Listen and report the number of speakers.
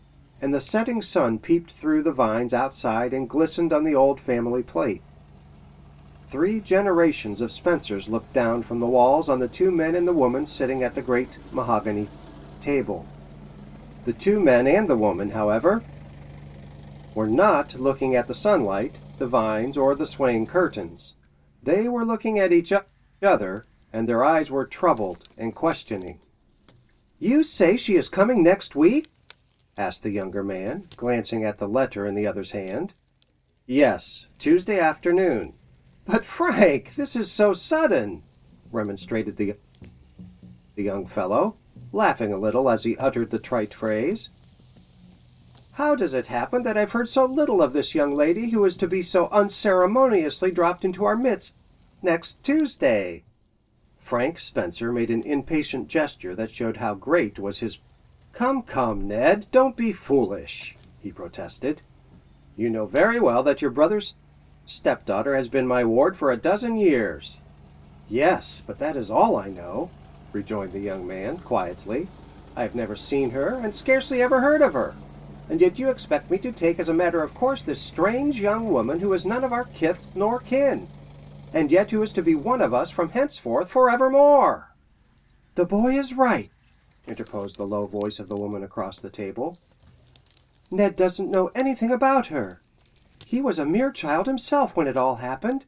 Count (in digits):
1